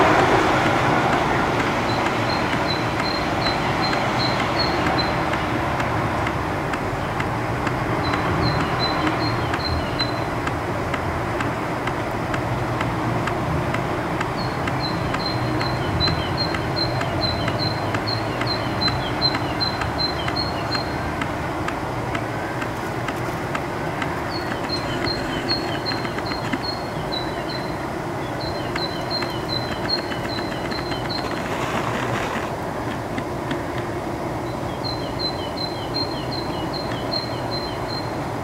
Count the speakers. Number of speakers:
0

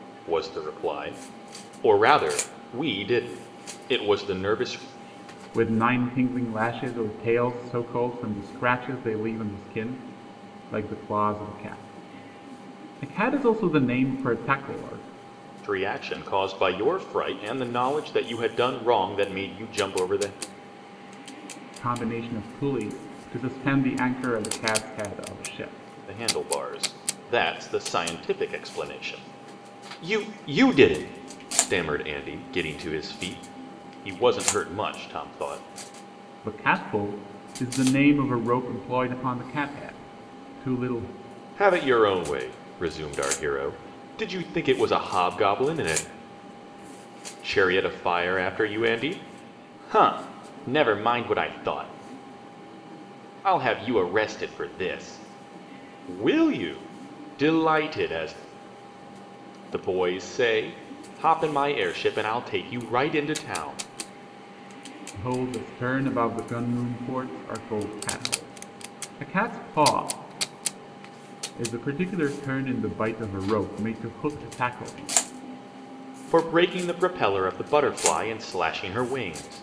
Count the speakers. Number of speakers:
2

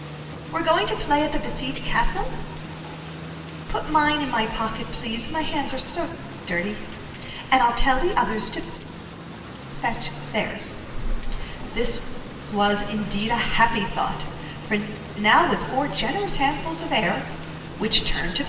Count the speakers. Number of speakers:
1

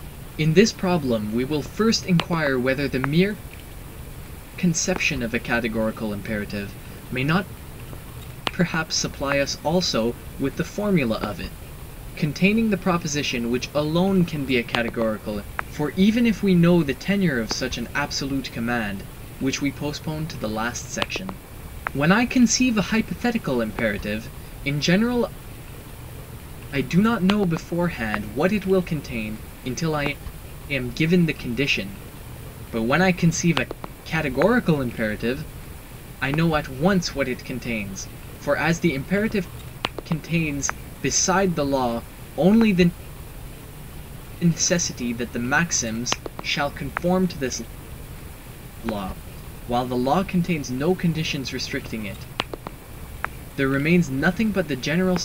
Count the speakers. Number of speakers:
1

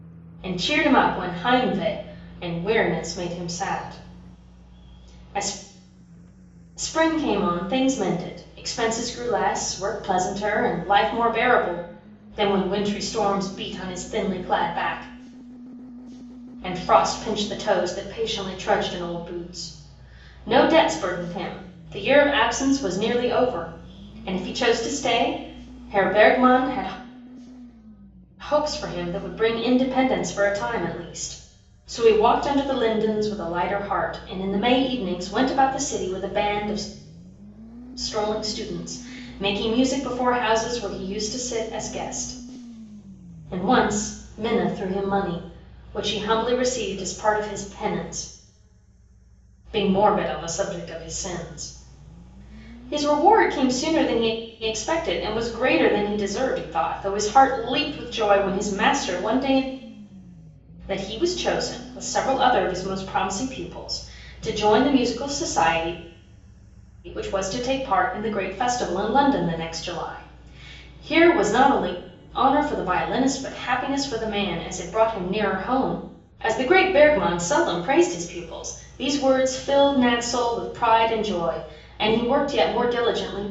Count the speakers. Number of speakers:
1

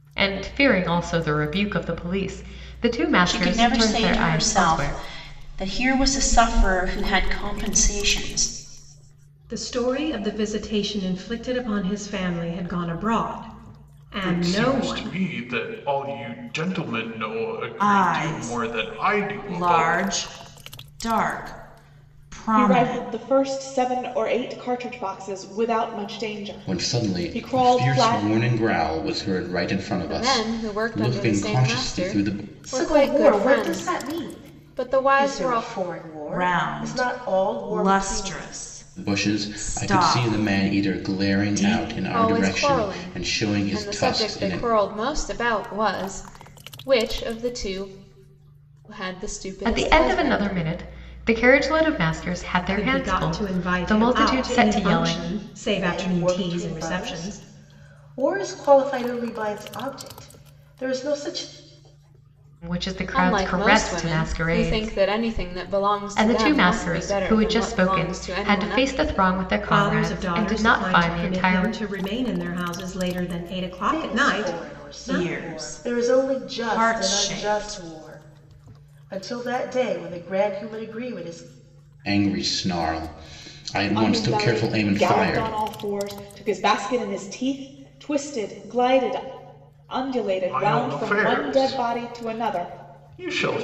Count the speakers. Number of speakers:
9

